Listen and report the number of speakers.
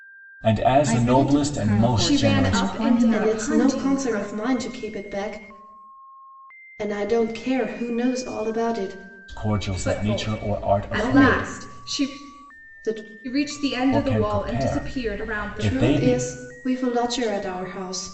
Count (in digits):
4